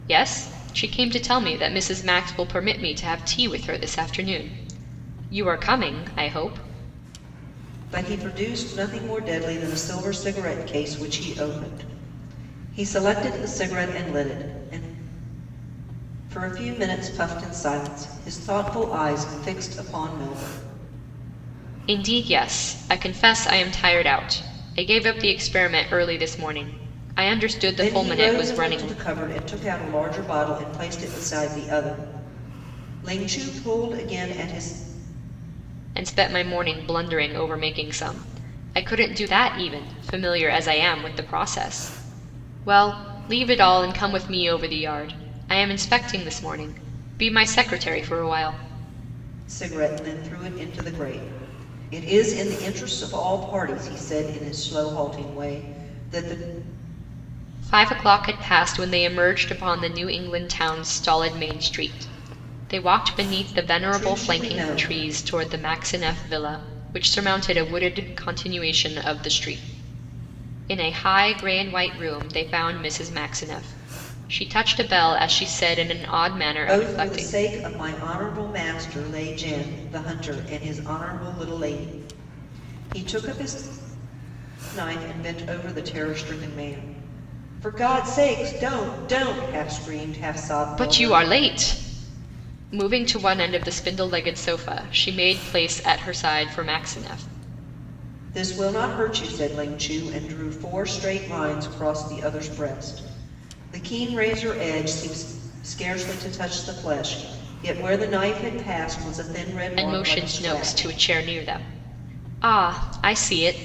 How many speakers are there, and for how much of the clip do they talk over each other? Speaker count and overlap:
two, about 4%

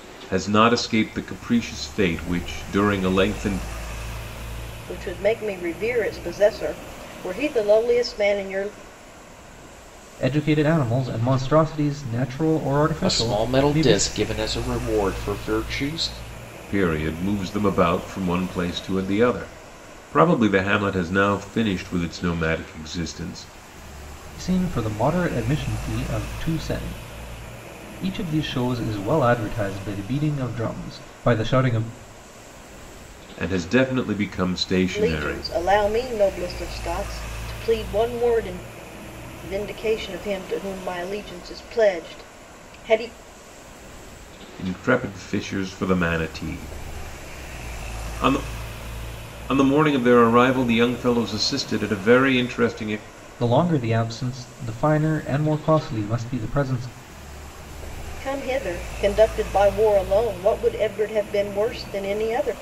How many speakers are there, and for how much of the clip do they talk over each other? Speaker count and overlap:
four, about 2%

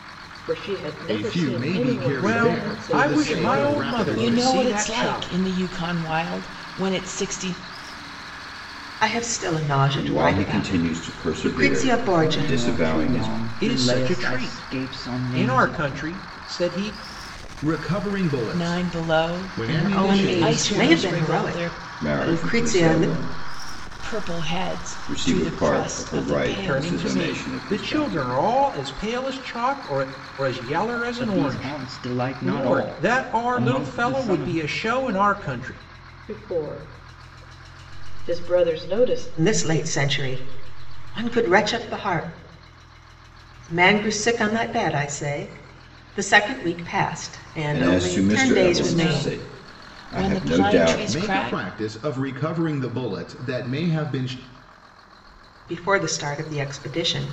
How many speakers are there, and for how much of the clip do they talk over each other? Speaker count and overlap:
eight, about 53%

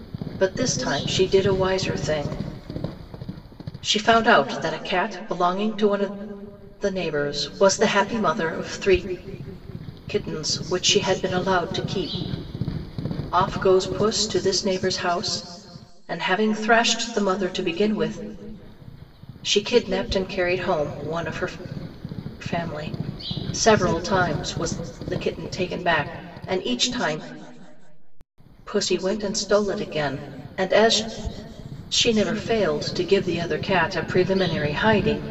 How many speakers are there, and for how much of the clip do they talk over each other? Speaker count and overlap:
one, no overlap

